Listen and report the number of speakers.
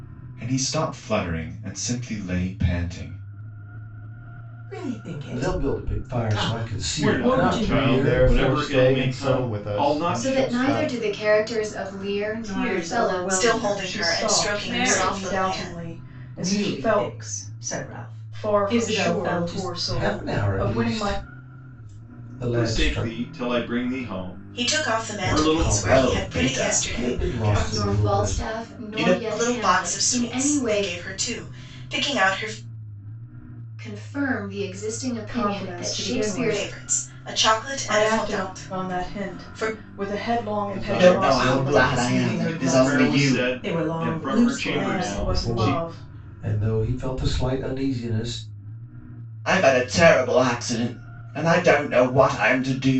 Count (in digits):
9